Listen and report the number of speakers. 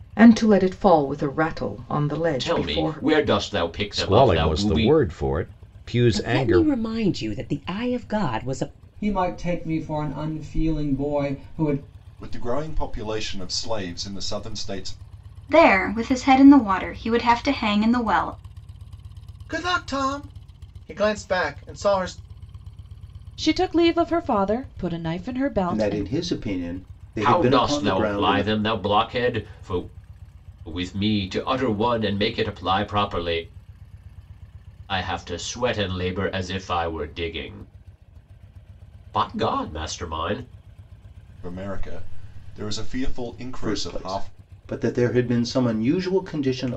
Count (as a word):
ten